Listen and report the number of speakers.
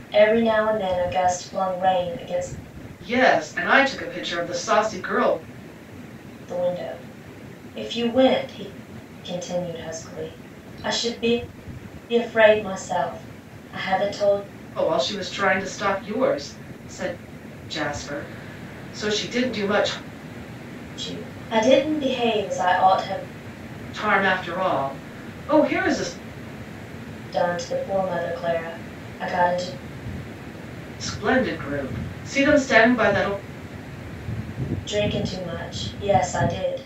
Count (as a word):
two